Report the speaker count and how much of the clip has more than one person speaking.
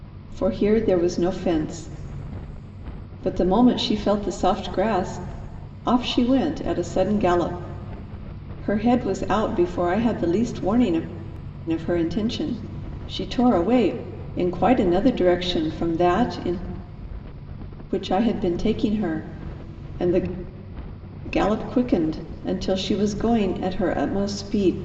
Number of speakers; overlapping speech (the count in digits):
1, no overlap